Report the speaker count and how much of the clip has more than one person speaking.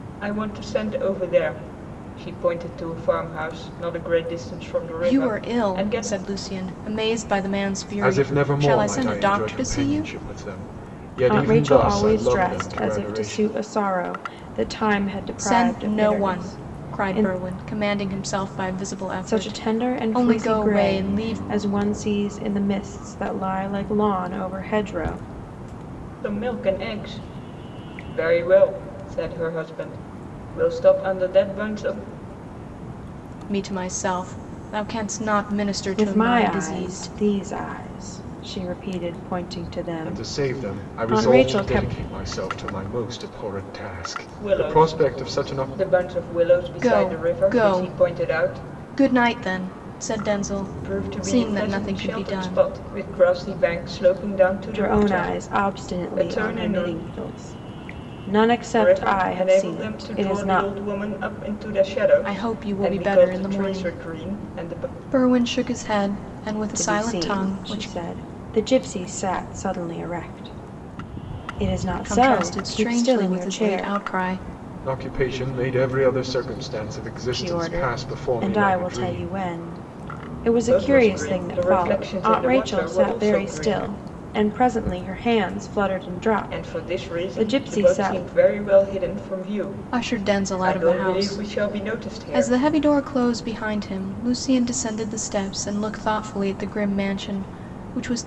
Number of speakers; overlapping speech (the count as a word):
four, about 39%